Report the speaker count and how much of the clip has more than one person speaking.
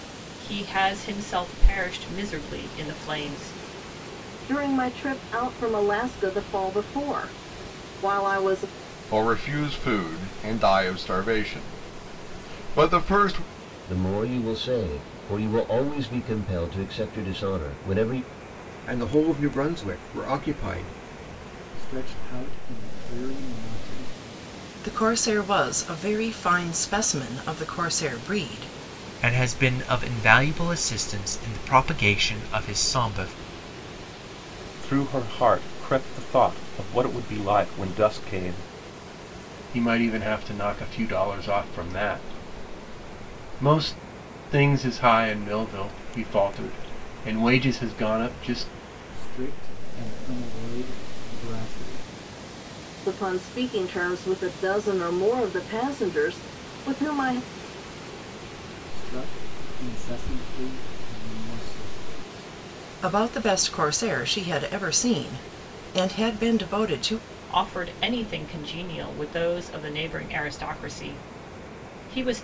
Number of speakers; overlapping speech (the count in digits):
10, no overlap